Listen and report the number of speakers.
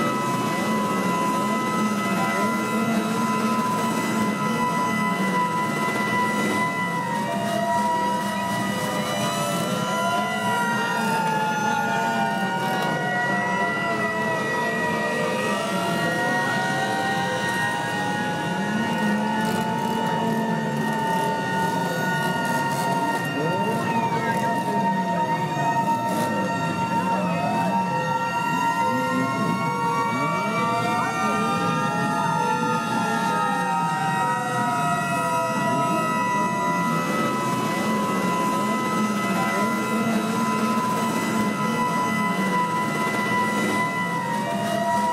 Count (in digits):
0